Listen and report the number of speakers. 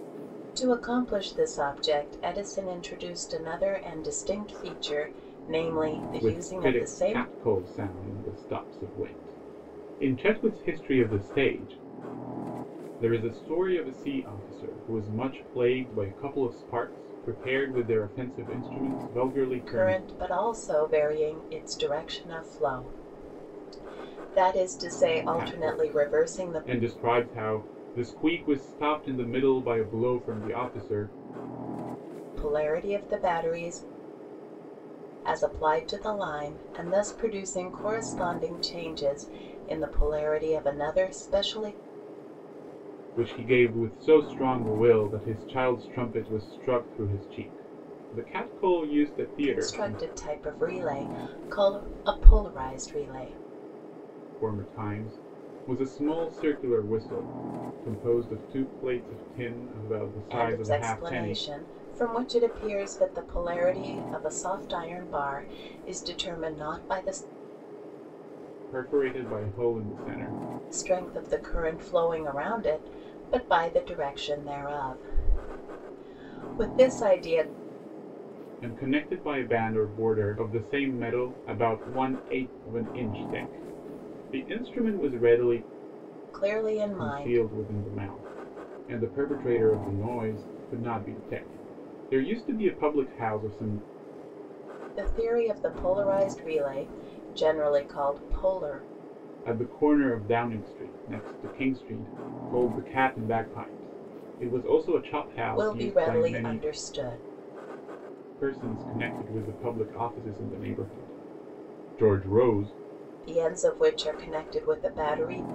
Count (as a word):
two